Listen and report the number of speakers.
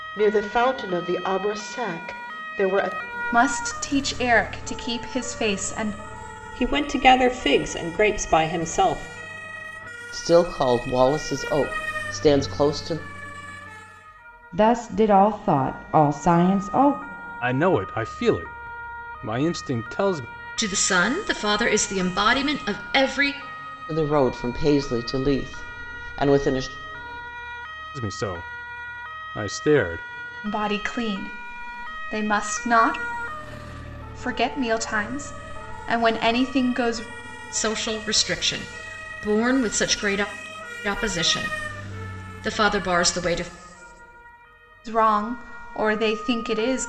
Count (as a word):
seven